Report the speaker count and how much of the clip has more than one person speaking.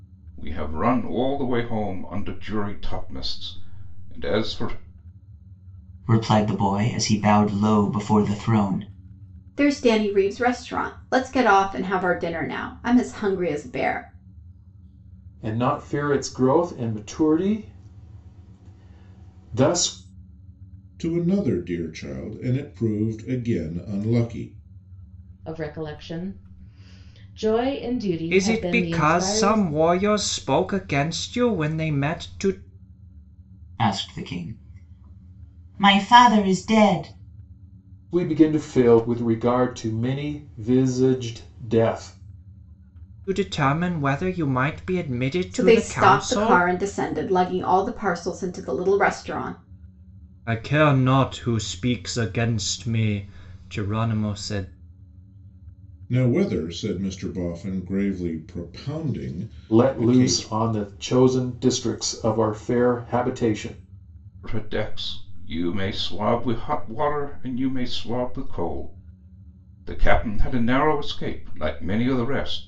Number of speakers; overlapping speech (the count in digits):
7, about 5%